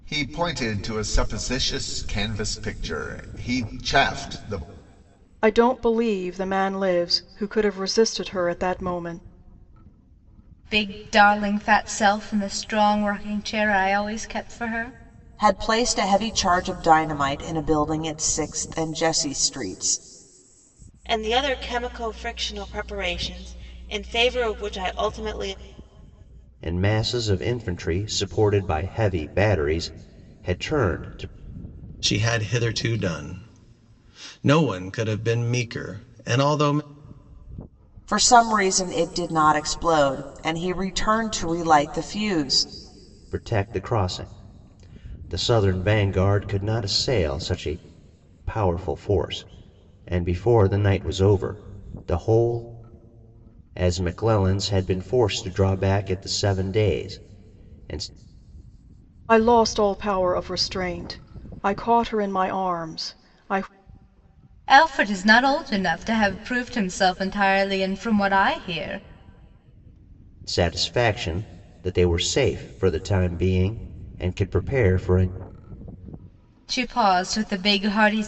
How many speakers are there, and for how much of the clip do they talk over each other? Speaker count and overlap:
7, no overlap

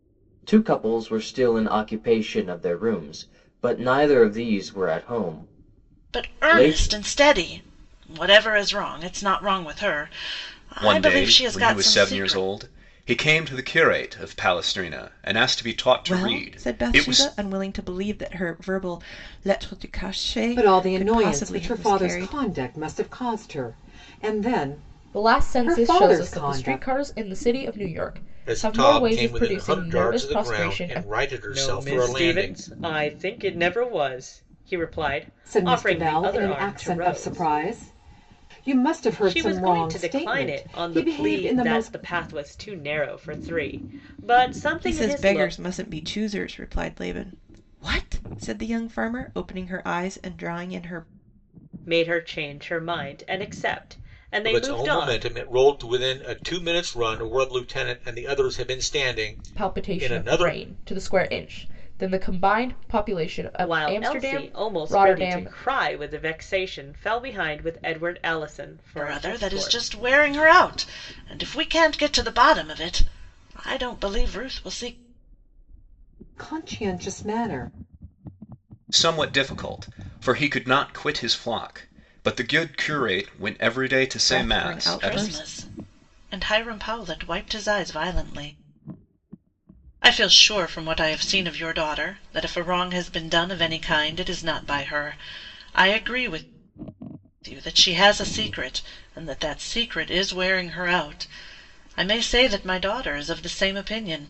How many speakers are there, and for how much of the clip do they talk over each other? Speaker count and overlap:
8, about 22%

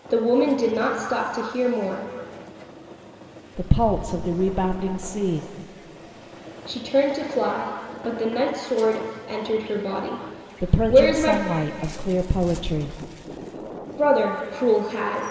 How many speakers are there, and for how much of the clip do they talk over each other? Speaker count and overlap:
2, about 6%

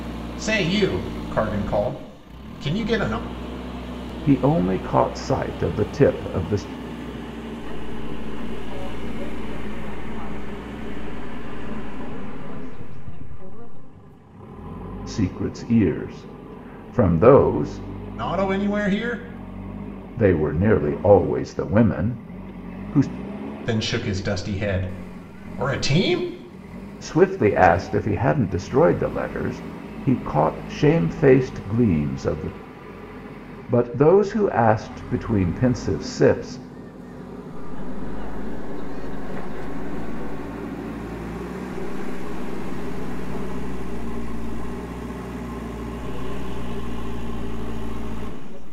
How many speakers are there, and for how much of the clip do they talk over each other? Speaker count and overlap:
3, no overlap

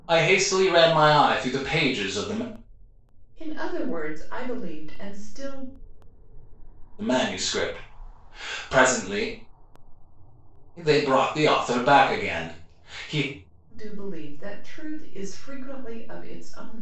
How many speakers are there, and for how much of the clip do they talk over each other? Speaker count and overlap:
2, no overlap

